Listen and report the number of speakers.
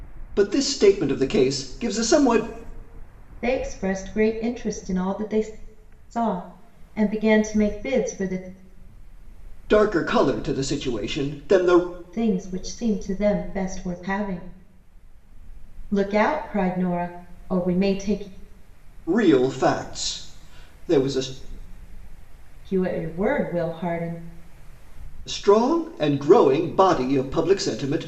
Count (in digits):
2